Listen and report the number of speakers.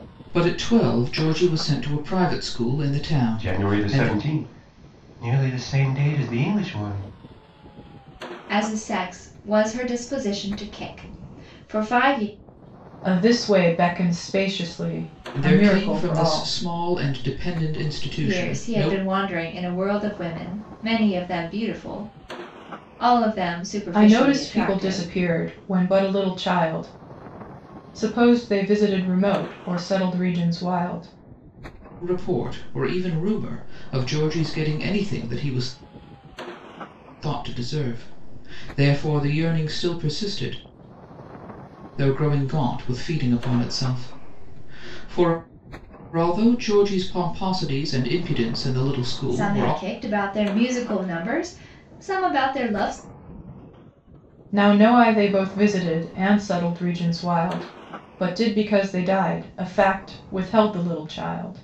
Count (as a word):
four